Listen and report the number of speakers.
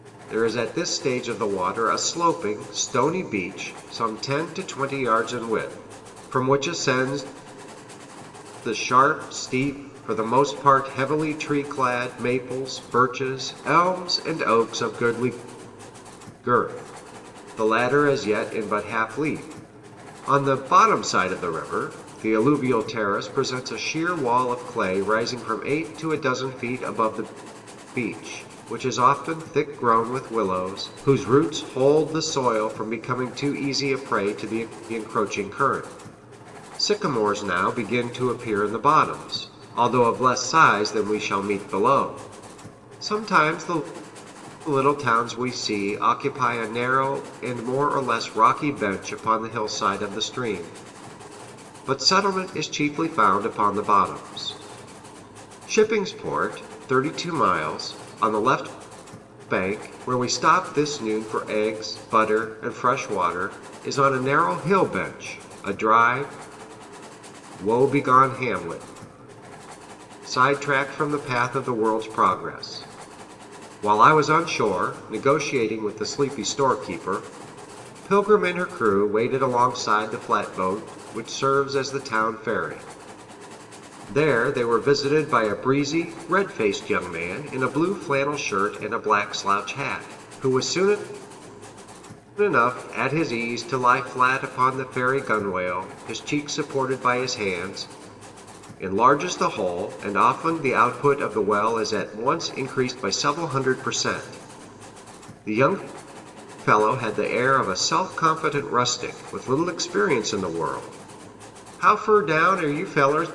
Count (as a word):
one